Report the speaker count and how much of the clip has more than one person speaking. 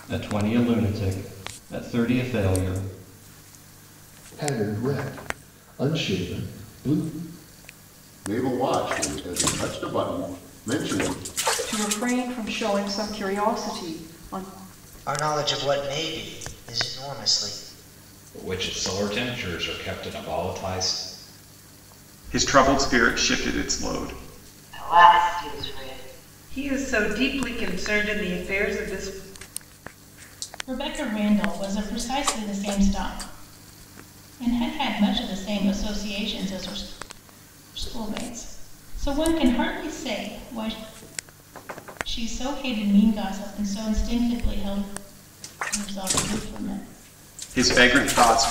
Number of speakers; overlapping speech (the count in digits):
10, no overlap